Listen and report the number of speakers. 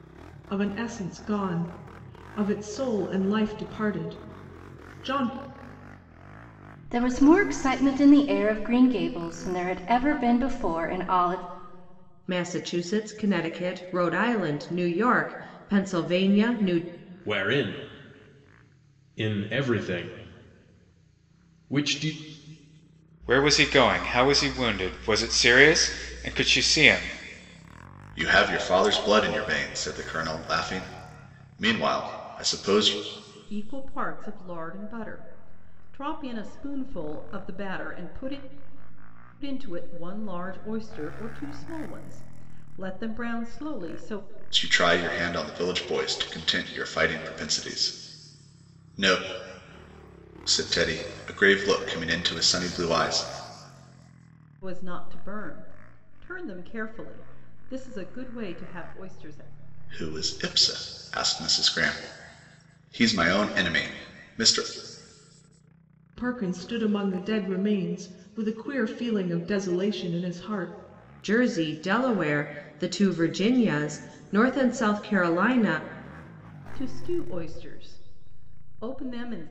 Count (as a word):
seven